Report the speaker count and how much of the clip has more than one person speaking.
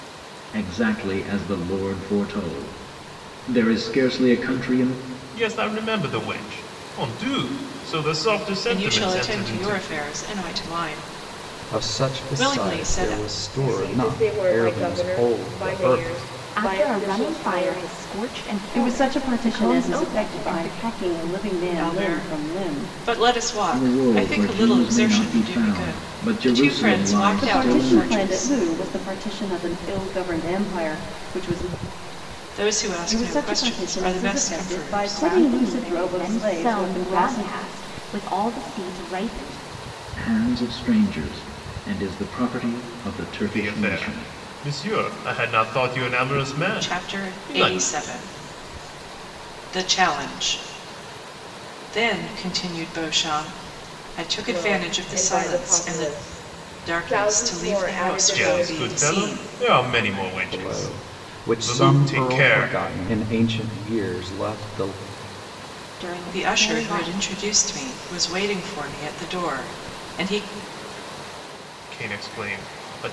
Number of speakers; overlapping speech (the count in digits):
7, about 39%